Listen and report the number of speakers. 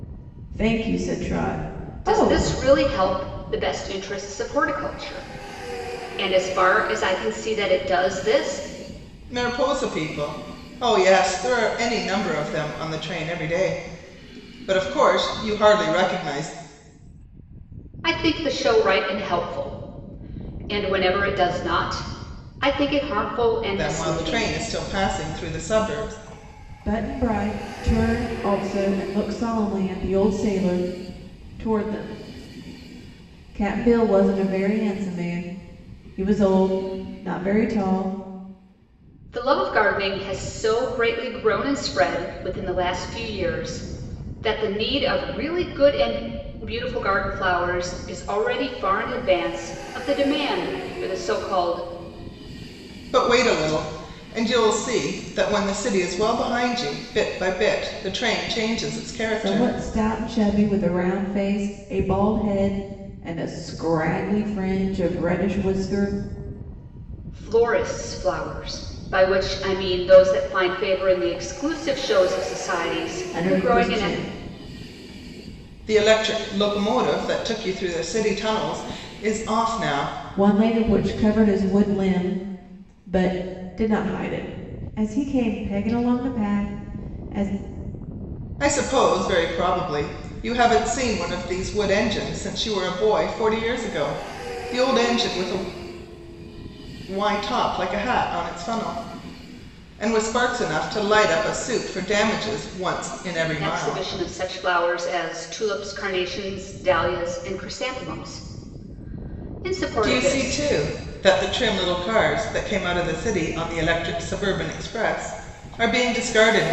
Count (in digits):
3